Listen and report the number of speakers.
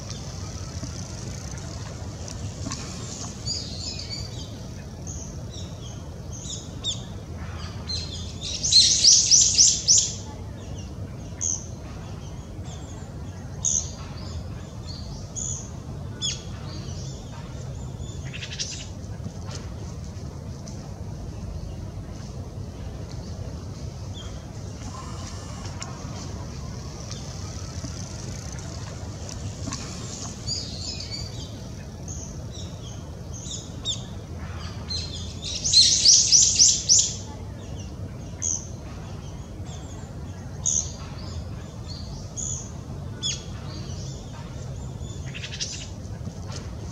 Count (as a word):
zero